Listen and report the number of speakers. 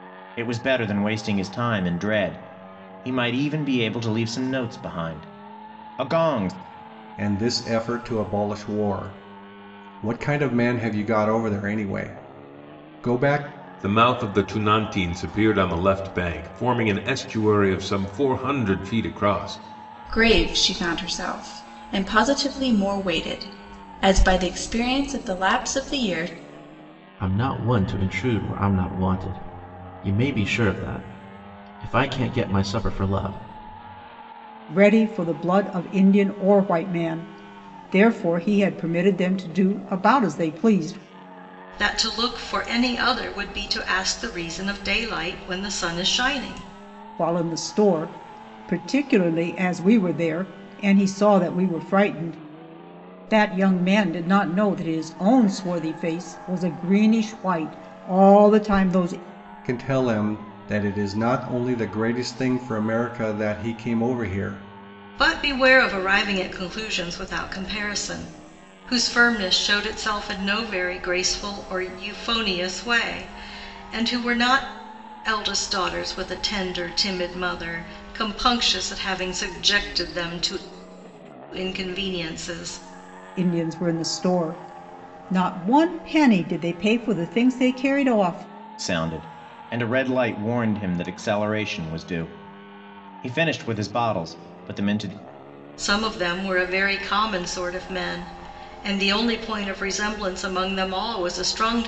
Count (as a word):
seven